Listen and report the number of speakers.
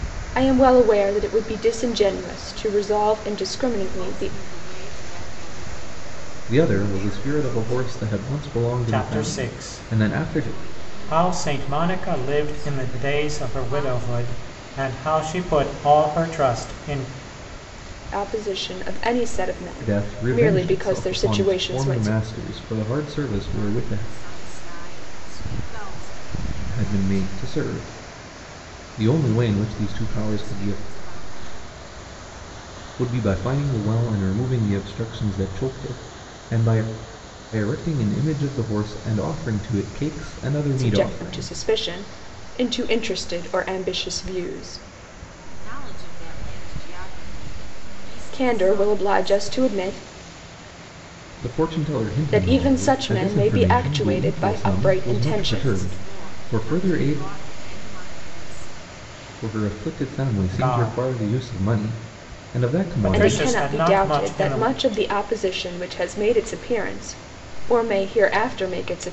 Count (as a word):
four